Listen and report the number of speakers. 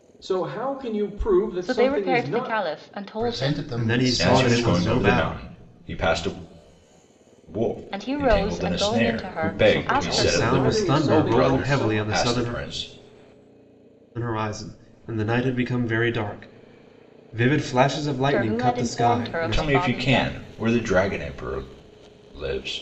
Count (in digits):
5